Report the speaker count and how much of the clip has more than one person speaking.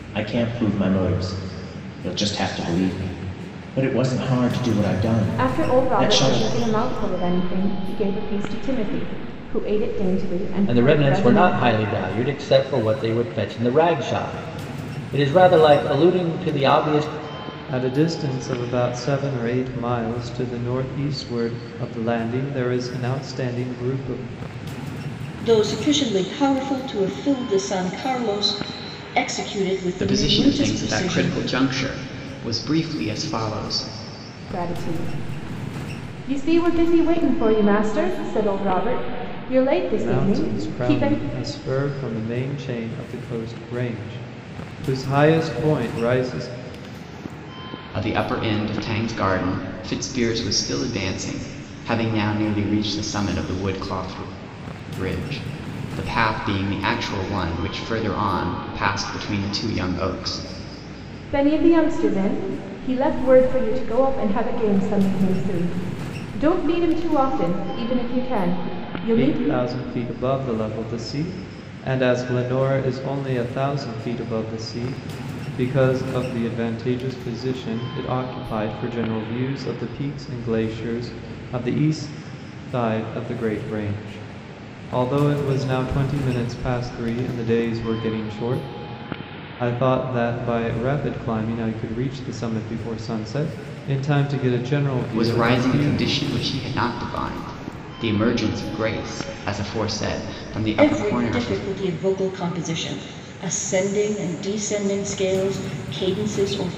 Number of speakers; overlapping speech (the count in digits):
6, about 6%